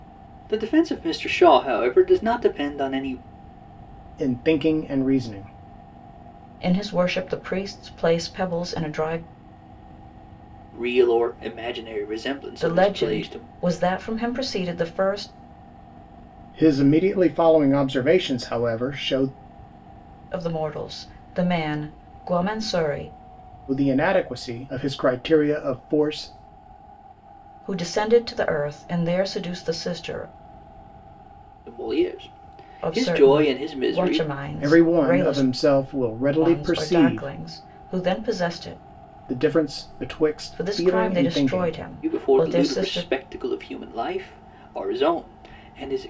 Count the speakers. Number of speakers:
3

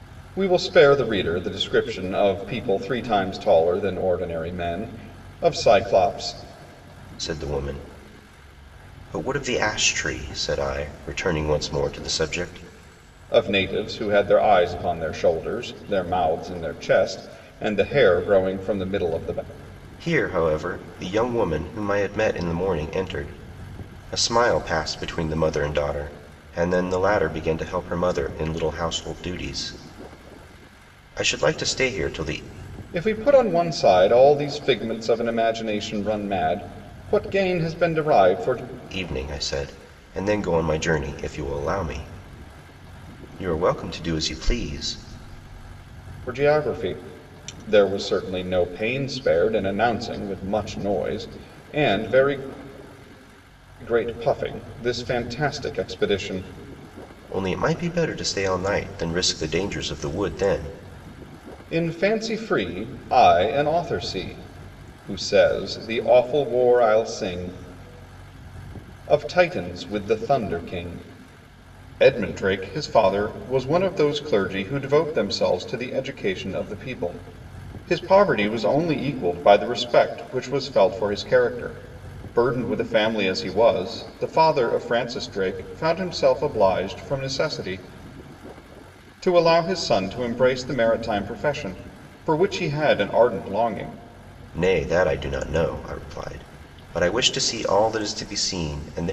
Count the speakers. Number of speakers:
2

